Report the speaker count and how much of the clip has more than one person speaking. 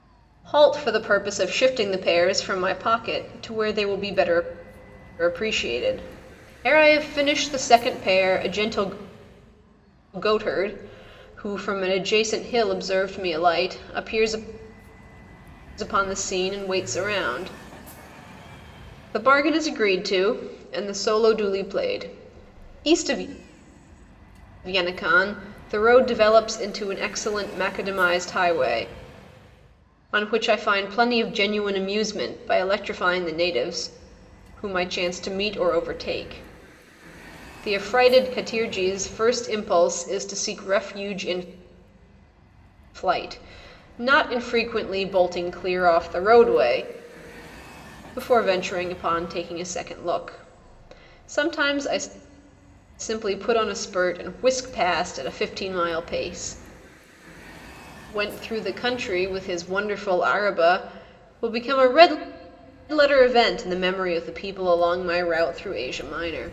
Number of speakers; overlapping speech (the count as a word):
one, no overlap